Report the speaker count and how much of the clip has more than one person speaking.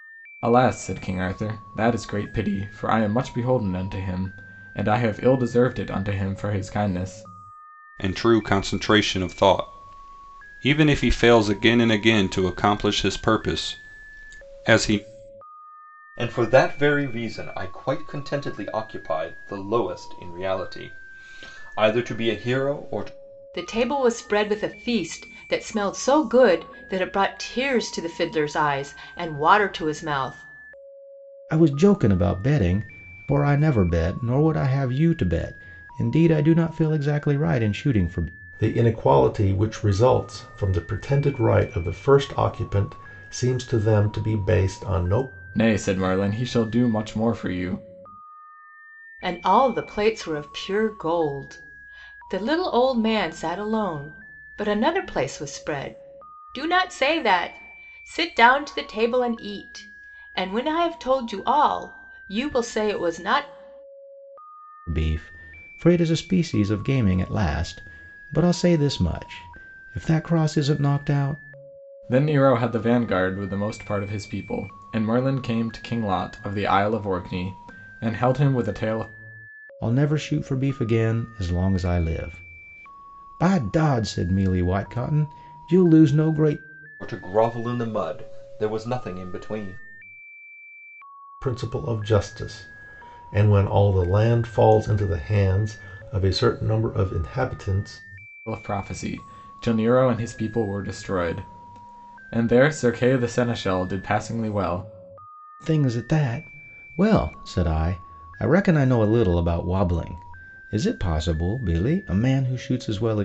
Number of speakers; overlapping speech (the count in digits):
6, no overlap